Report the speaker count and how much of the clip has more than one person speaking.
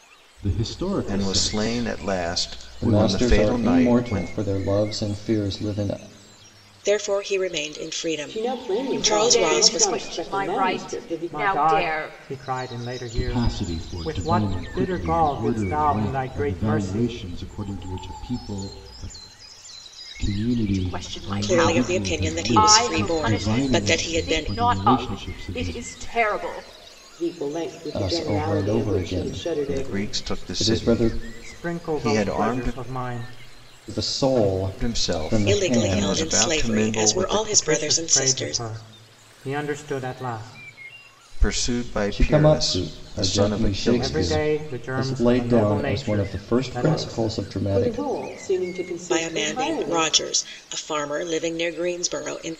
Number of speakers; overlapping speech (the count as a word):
seven, about 61%